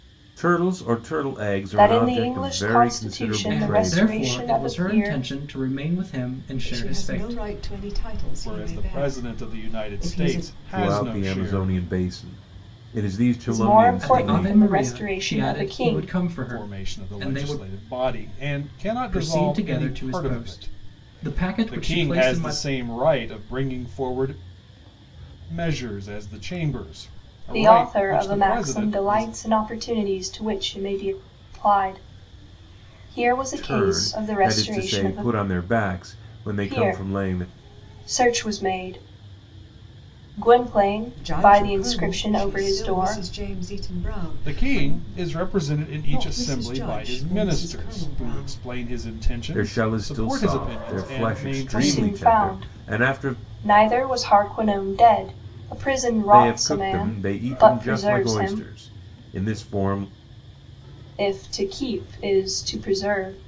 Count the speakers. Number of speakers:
5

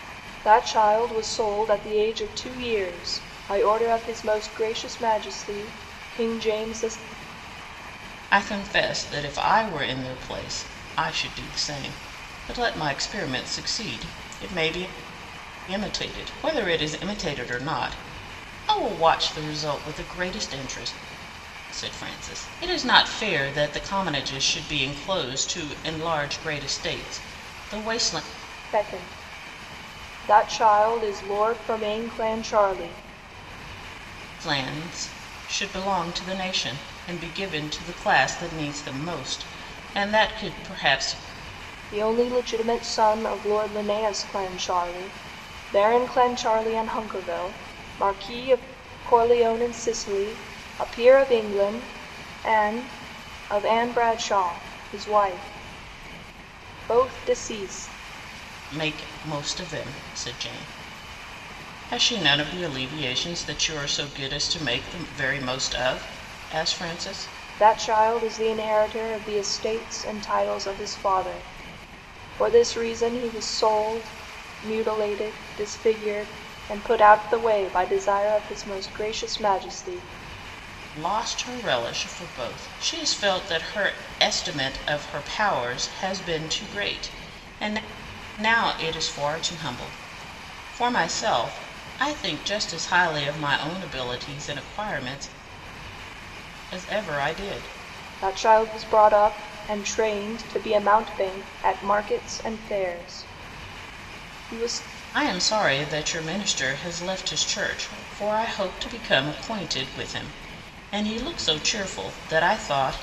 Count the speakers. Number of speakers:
2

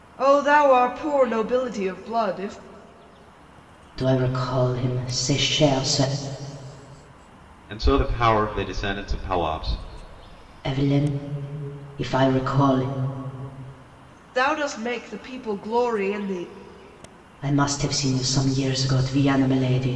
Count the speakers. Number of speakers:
3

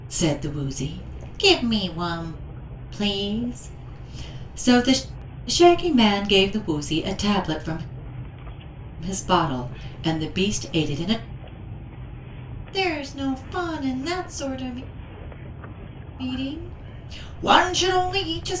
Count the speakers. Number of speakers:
1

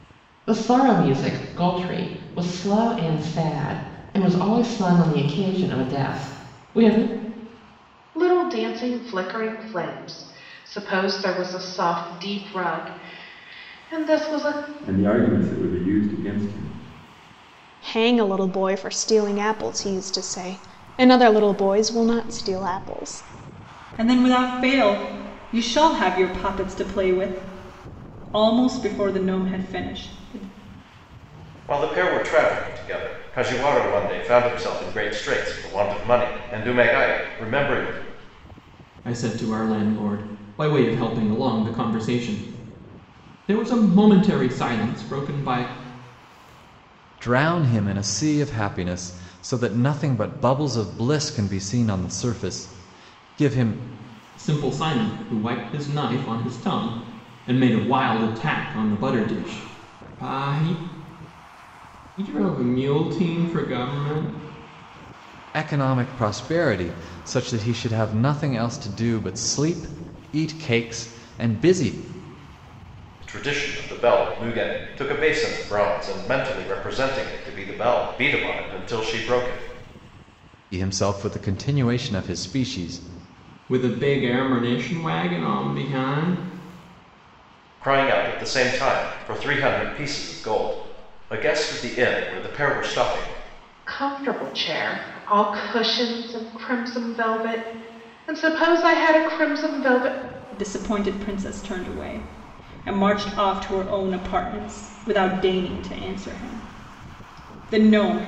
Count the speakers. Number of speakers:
8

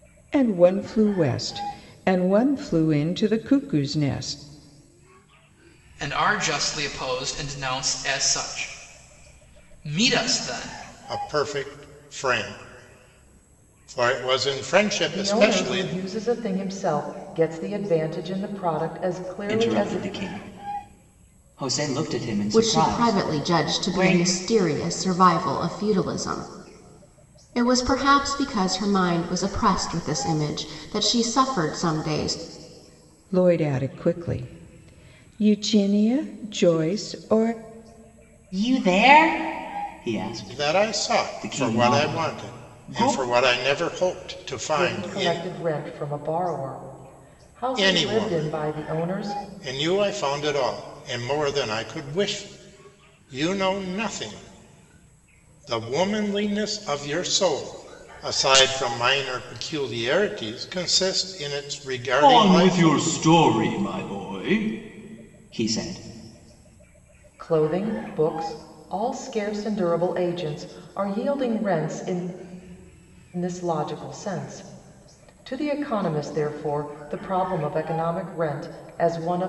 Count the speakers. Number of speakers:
6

